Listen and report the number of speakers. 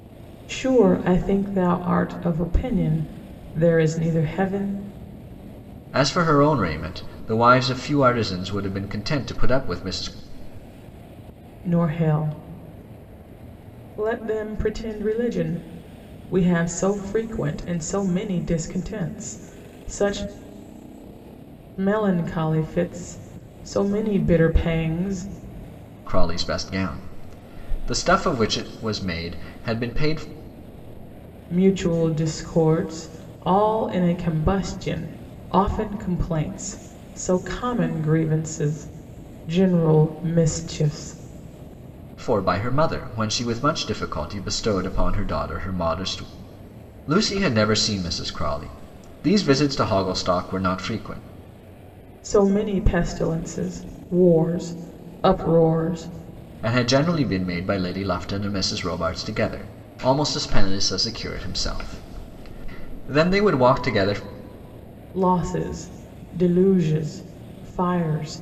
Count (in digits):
2